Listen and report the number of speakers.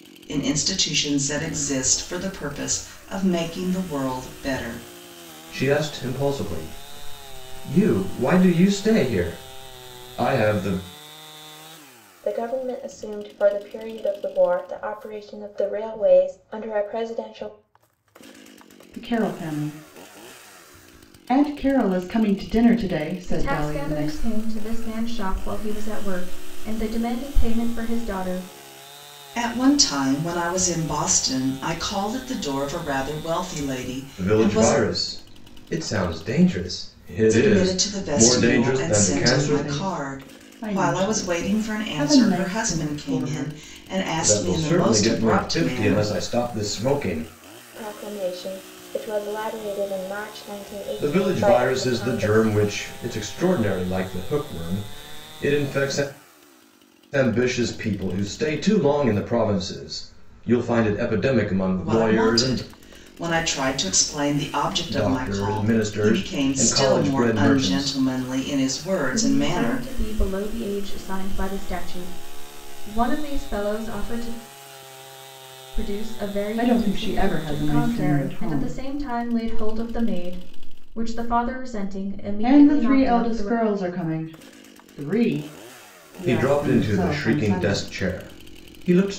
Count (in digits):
5